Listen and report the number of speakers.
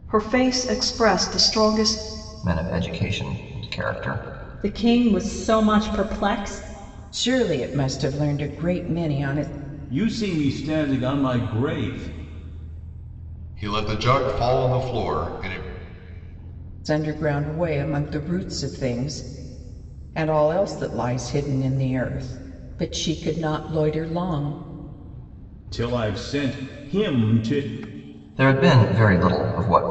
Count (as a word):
six